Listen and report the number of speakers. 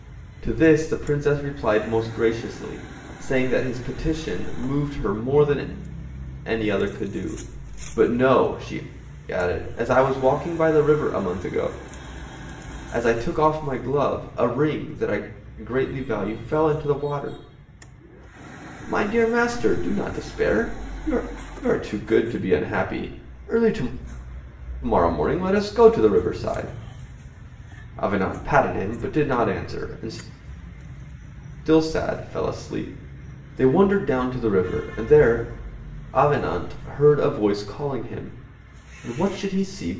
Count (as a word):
one